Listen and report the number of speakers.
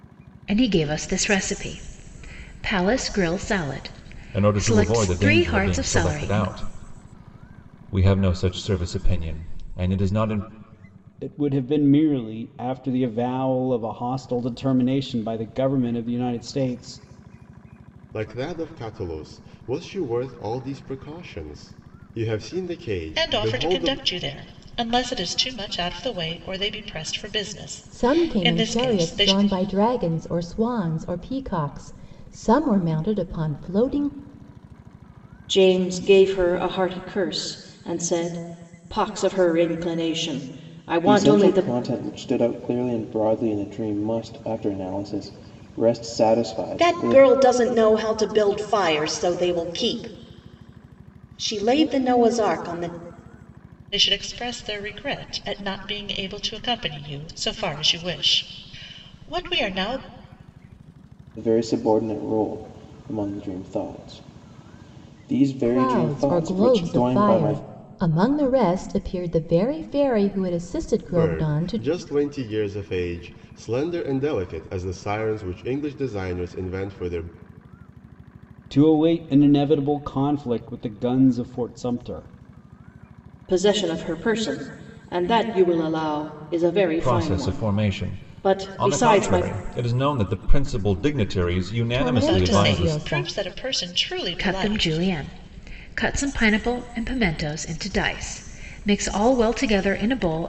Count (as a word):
nine